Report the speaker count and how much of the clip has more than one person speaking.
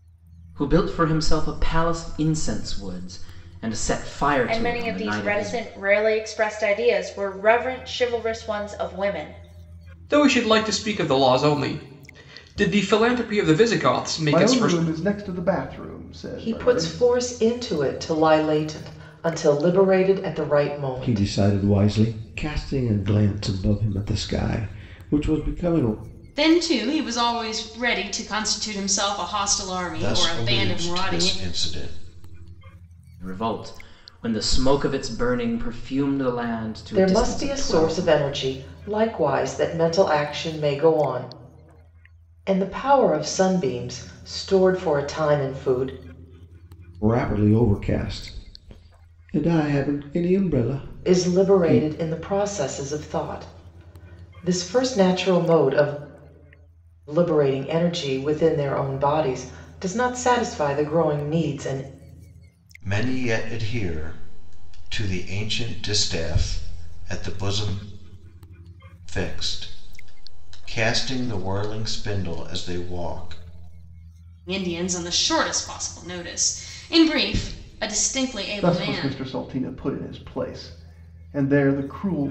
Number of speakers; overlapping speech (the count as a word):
eight, about 8%